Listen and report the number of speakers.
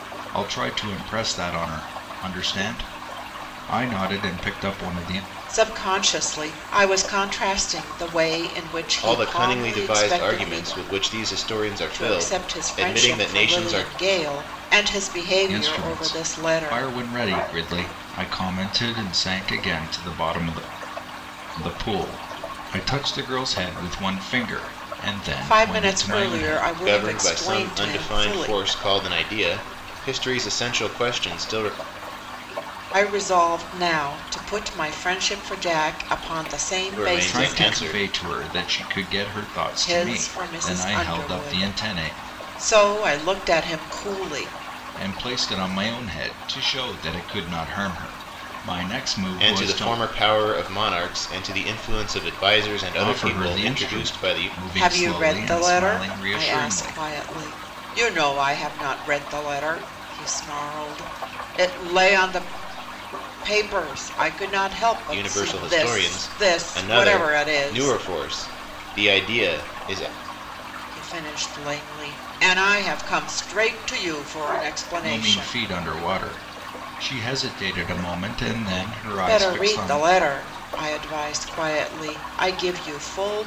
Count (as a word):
three